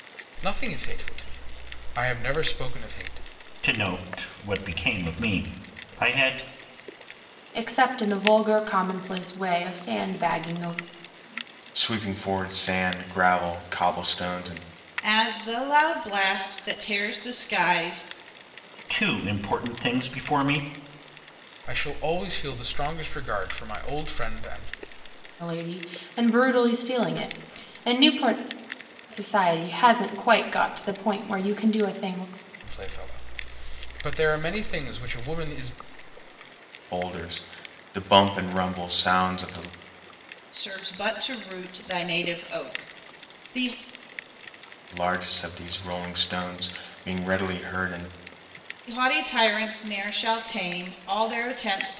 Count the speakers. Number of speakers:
5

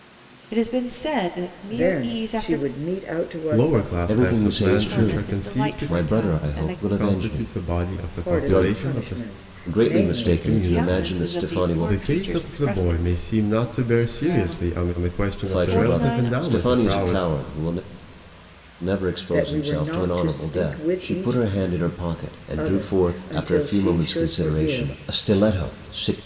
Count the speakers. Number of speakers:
4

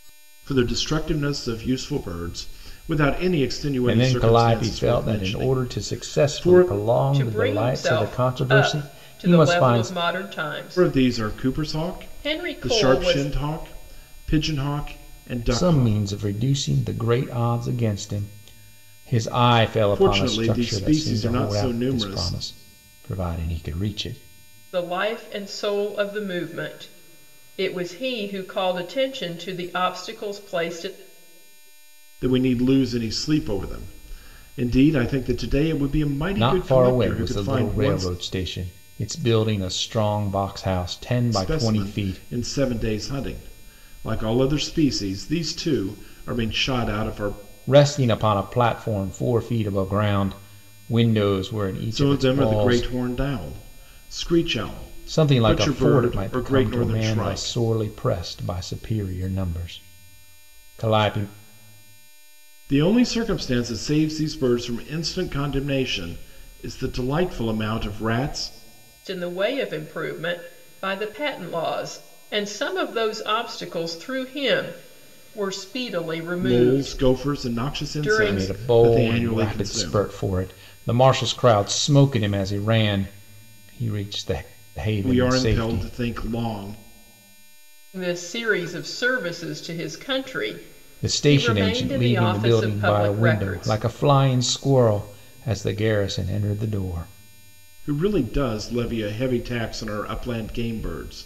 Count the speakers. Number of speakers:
3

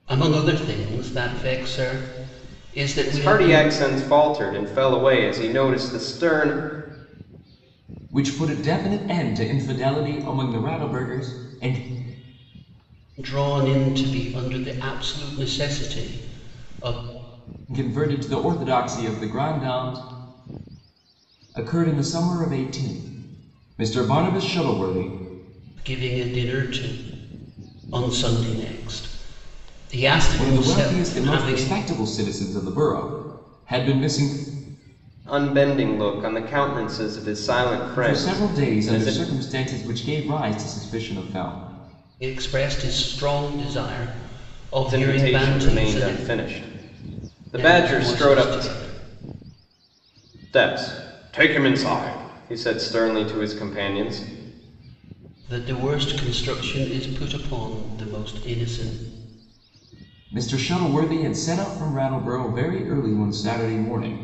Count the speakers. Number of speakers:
3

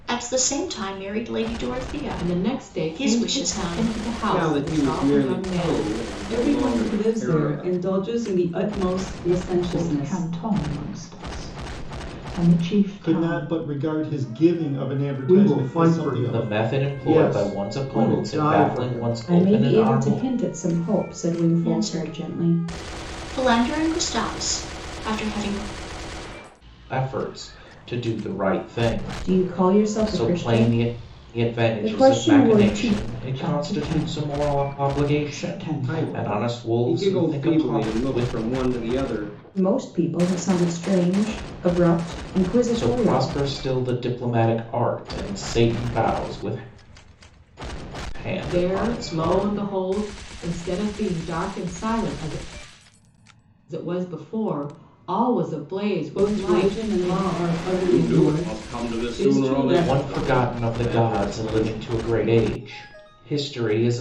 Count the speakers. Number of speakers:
9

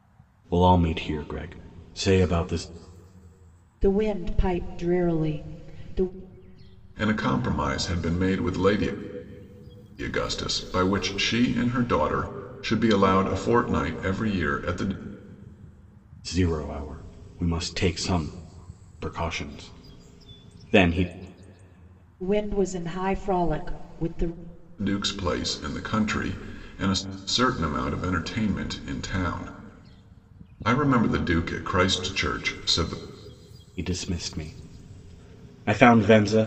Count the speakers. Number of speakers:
3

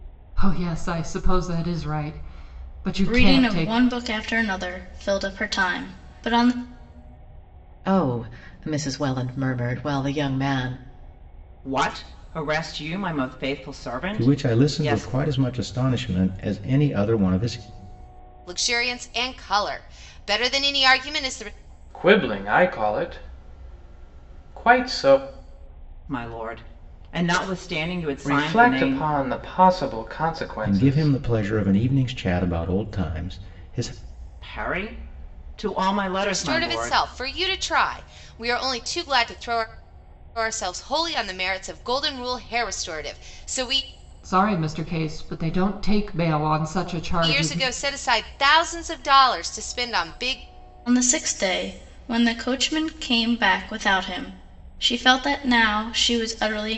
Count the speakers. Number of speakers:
7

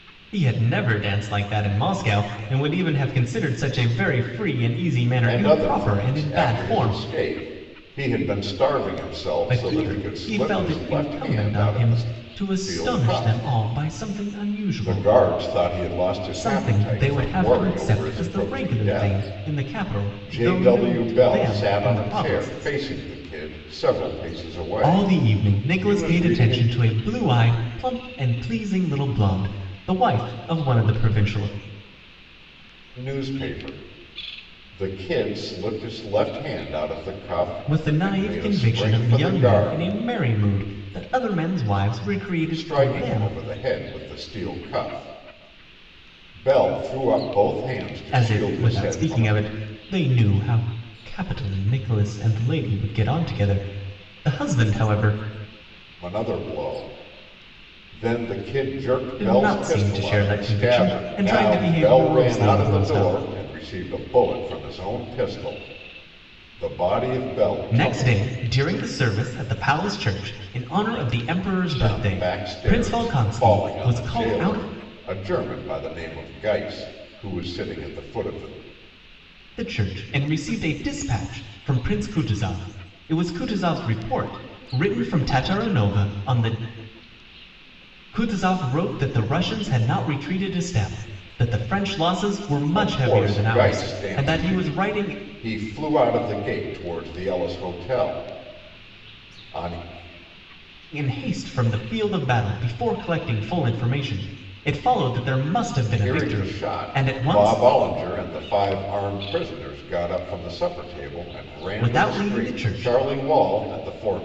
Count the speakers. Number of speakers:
2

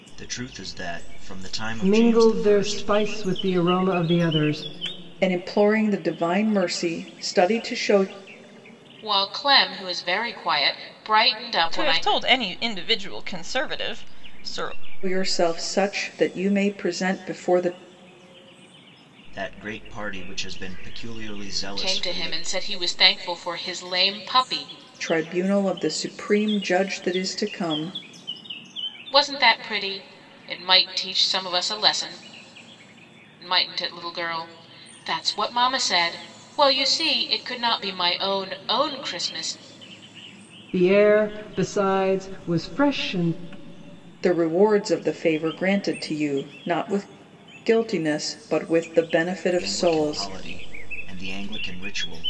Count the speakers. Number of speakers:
5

